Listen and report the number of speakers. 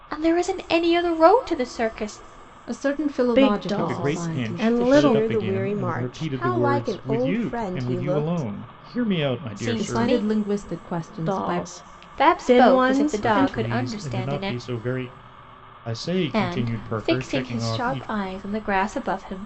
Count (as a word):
five